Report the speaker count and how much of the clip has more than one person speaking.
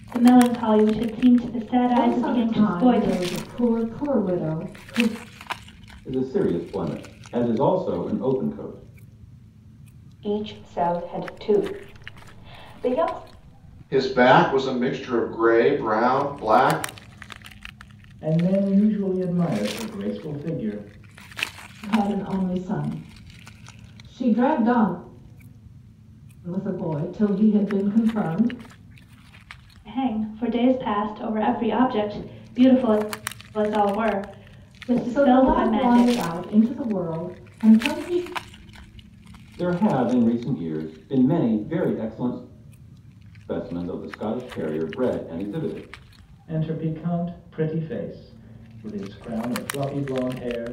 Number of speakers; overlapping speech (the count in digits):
6, about 5%